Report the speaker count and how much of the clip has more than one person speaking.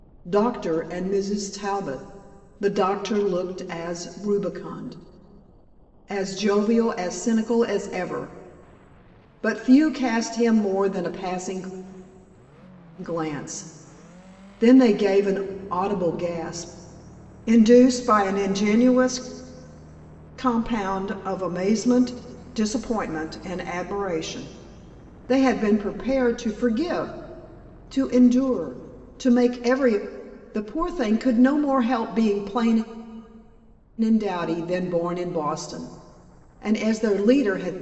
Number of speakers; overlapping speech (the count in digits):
1, no overlap